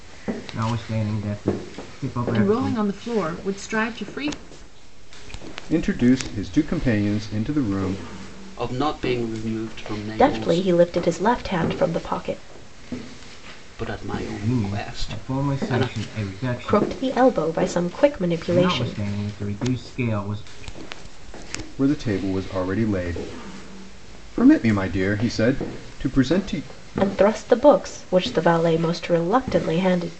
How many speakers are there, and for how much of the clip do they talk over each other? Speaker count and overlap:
five, about 11%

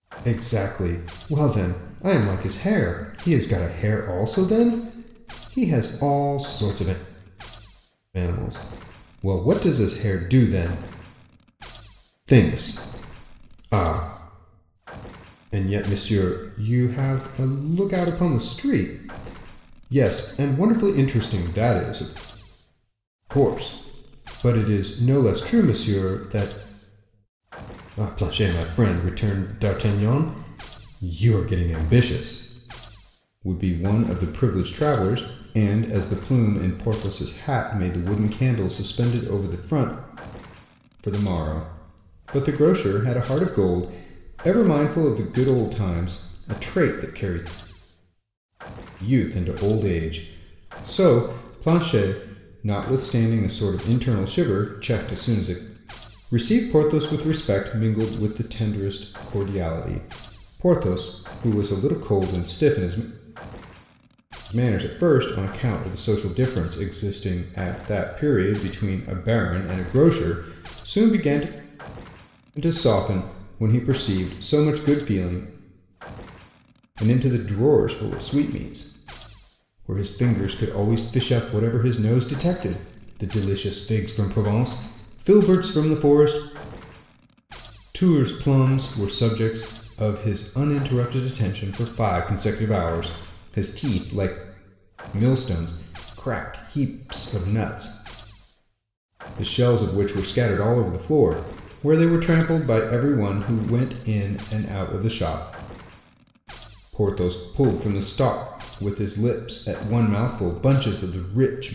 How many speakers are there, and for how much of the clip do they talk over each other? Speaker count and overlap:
one, no overlap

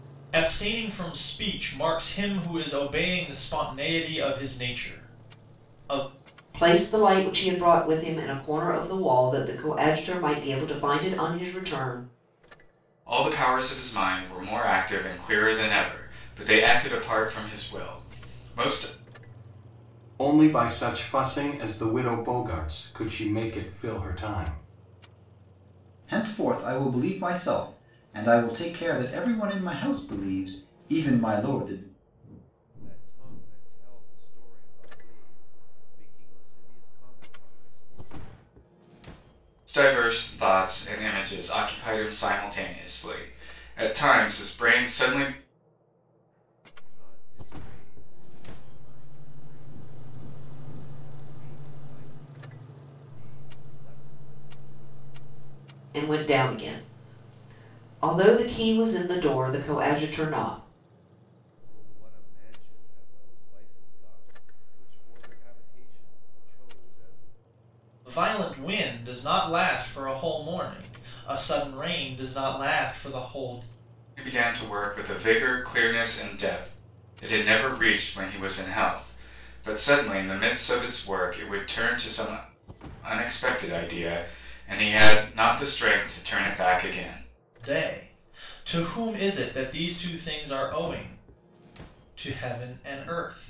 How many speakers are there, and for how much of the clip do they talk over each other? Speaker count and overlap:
six, no overlap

